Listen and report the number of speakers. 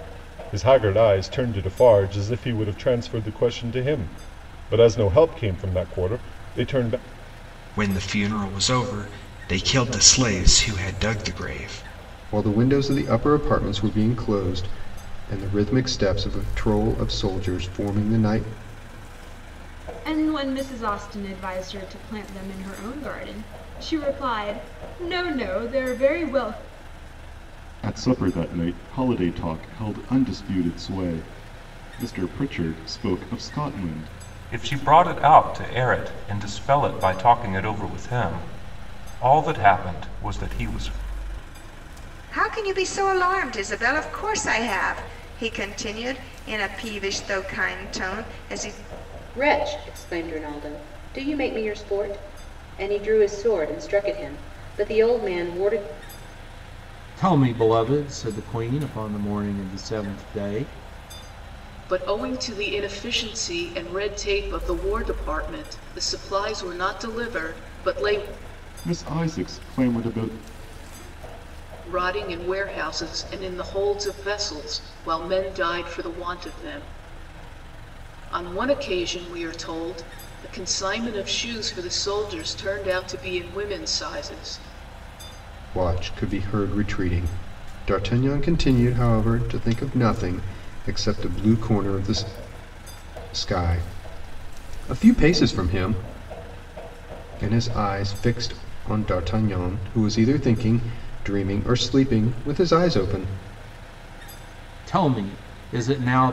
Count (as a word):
ten